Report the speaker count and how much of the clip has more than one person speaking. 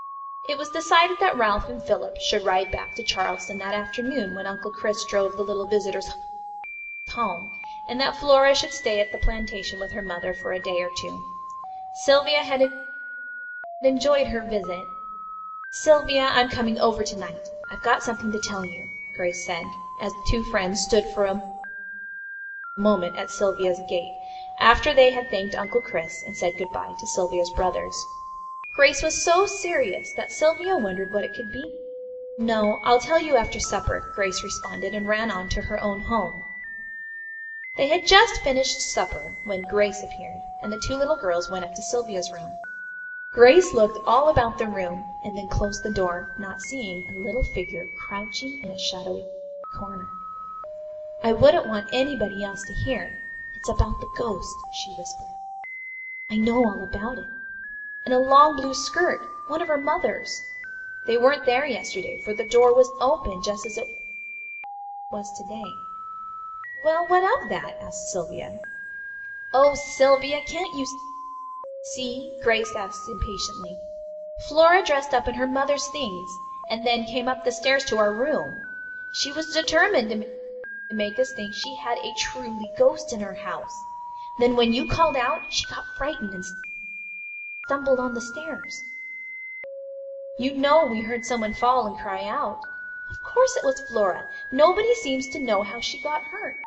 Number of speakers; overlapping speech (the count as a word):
one, no overlap